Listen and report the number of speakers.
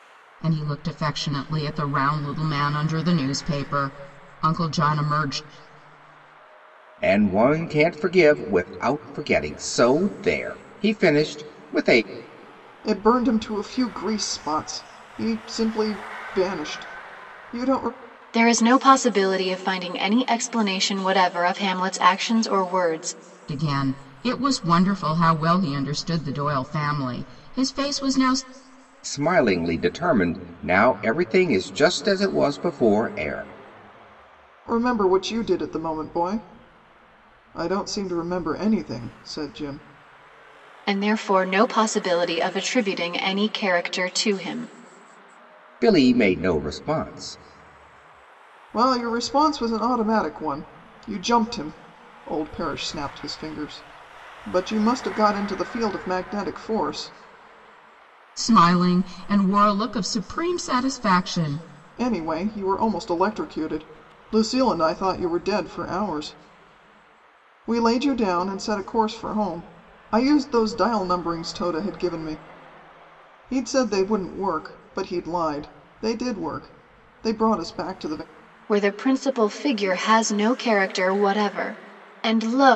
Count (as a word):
four